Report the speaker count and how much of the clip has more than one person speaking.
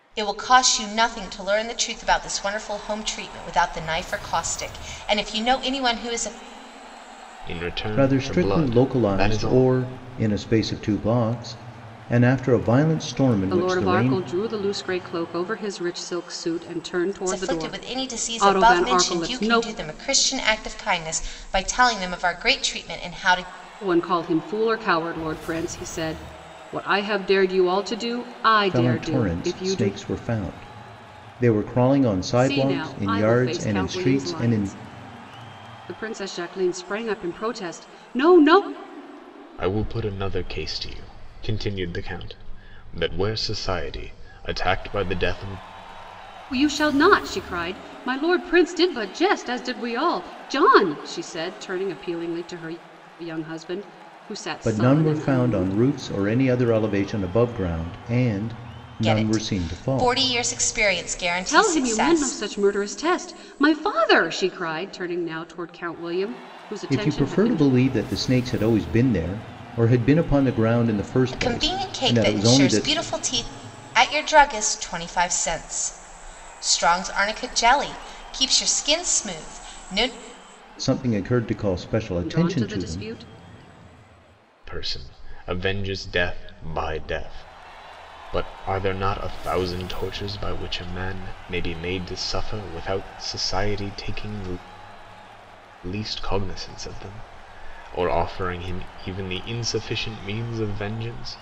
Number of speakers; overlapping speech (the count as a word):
four, about 15%